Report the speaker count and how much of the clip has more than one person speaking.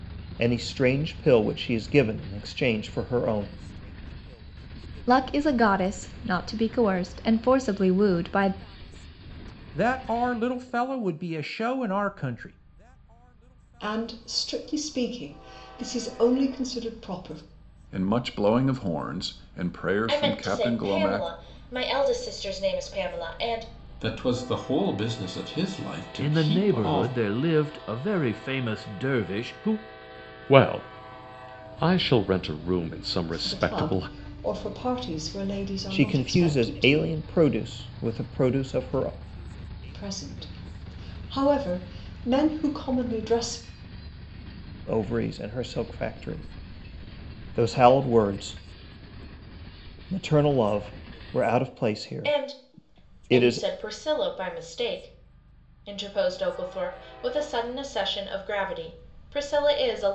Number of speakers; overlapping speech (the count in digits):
9, about 9%